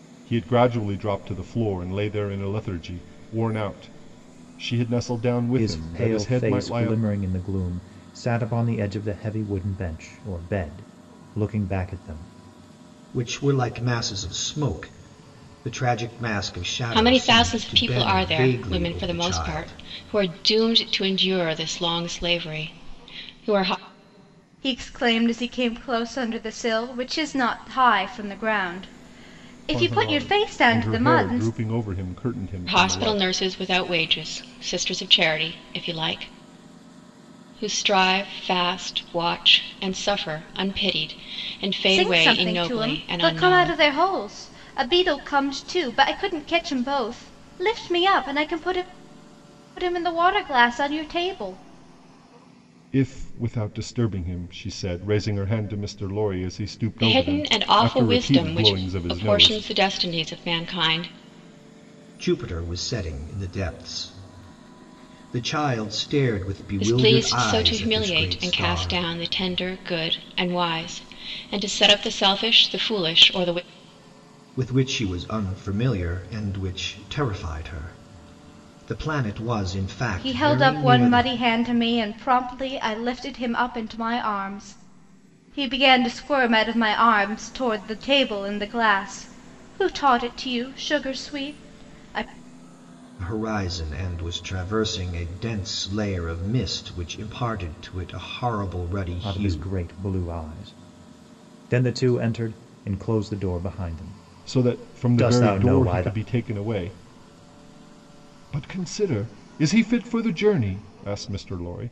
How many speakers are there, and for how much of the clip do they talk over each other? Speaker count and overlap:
5, about 16%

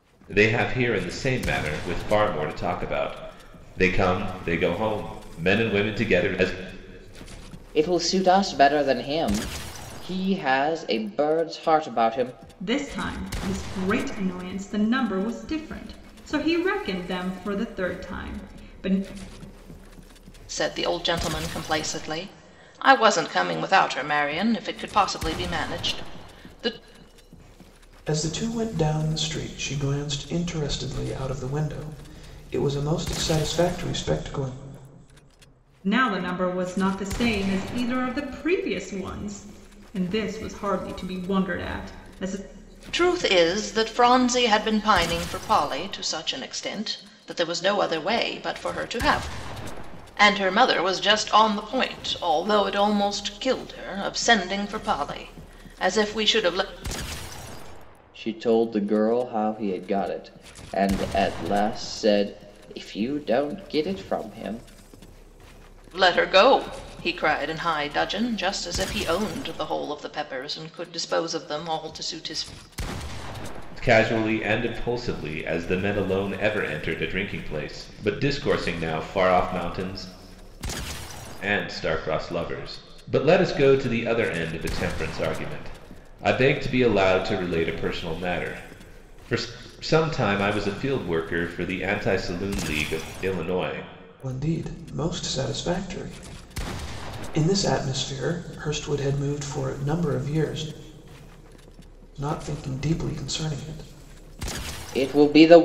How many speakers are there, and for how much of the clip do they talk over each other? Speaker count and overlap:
5, no overlap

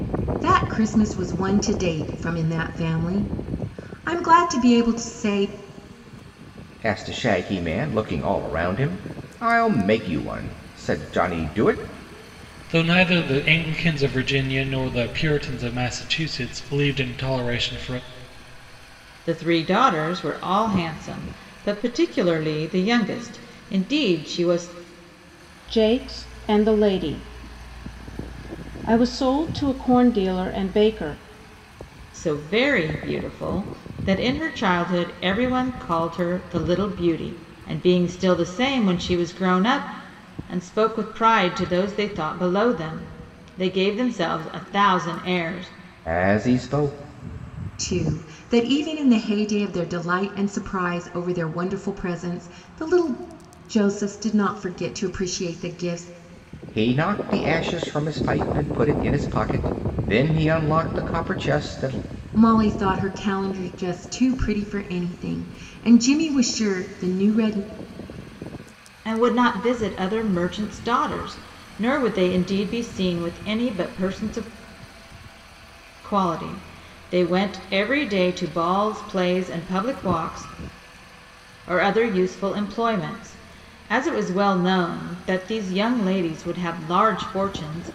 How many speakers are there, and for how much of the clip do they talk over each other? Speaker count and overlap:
5, no overlap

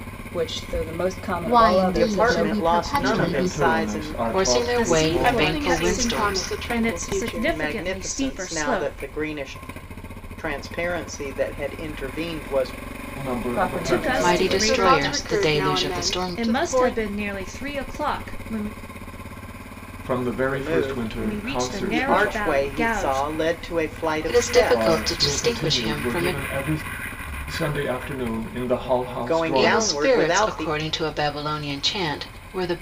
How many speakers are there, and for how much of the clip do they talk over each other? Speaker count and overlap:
7, about 54%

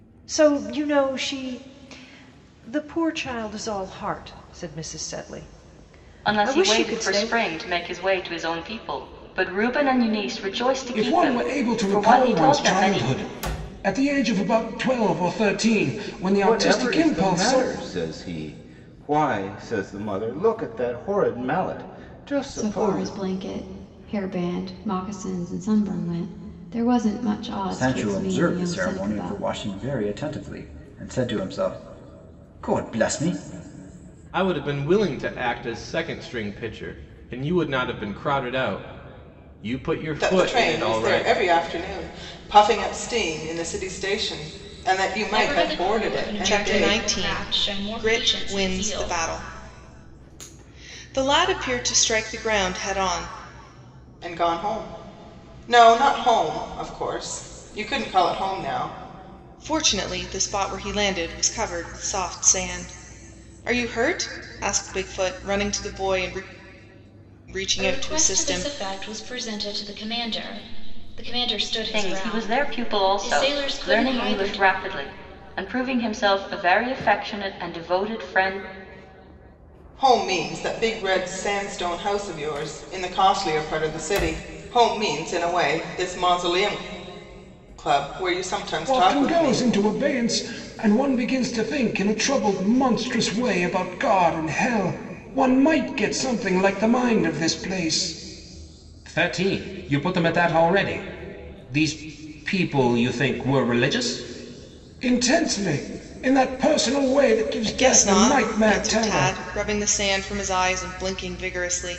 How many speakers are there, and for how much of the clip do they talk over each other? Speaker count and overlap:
10, about 17%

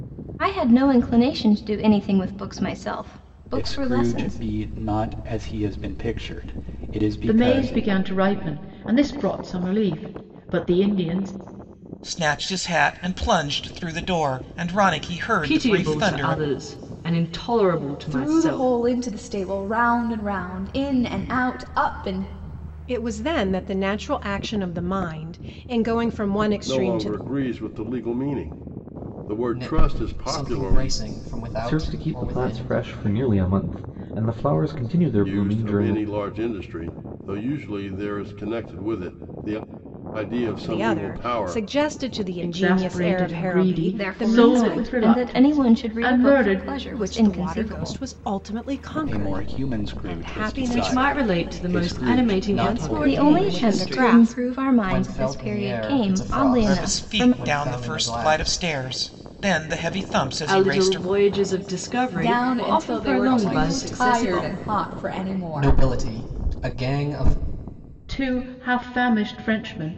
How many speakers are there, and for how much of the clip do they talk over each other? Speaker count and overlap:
10, about 39%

